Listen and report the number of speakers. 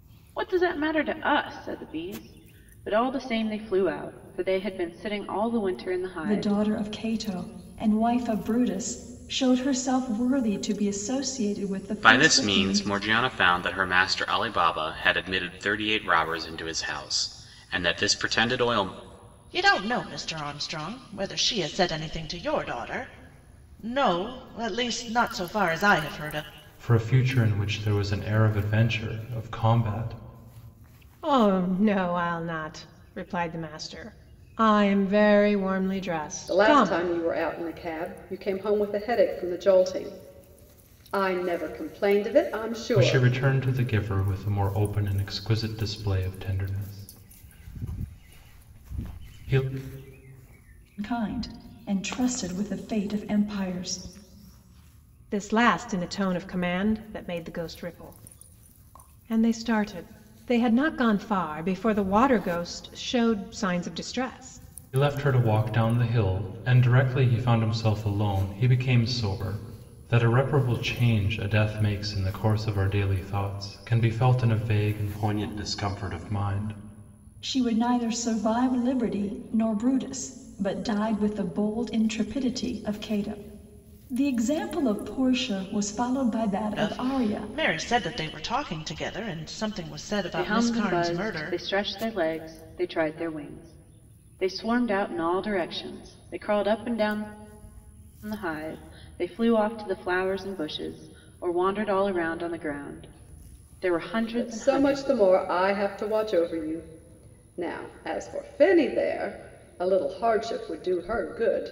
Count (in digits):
7